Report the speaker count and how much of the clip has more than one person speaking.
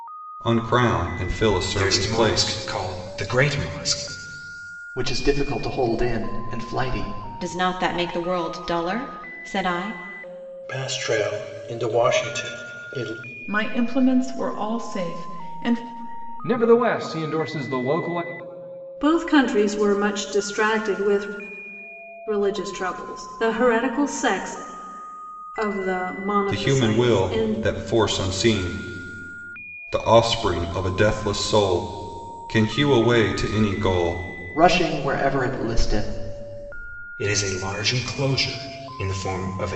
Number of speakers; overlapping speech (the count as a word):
eight, about 5%